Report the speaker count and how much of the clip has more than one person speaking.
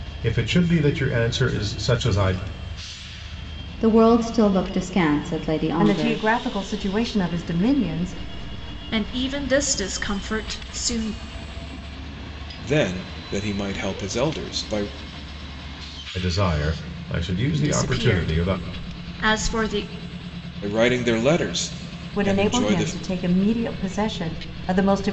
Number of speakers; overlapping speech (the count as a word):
five, about 9%